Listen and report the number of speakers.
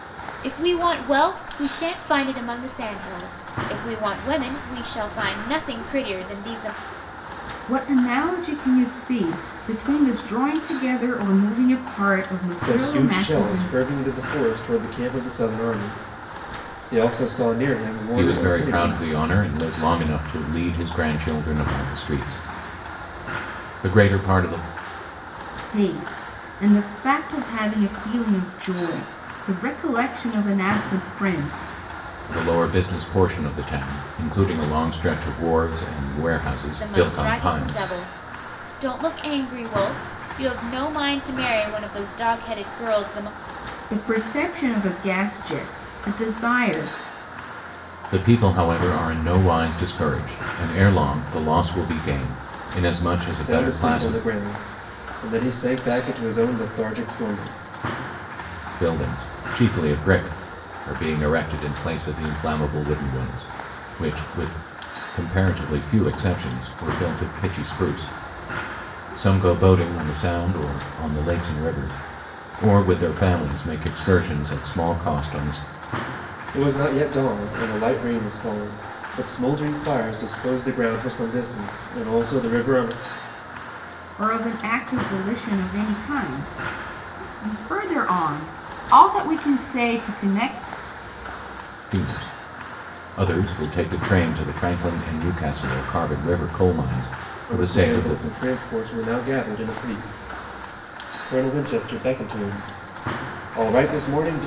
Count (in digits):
4